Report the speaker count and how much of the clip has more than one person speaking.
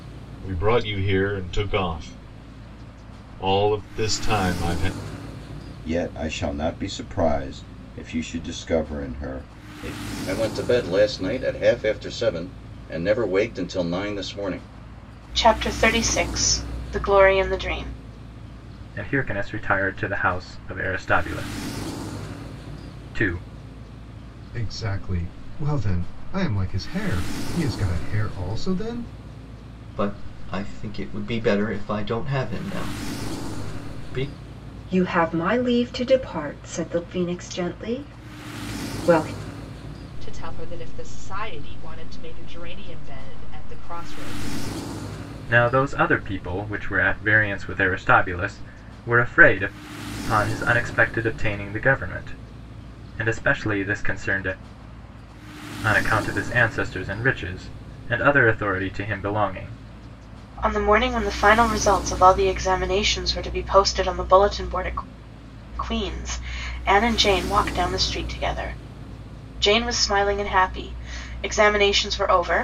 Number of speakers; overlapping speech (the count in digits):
9, no overlap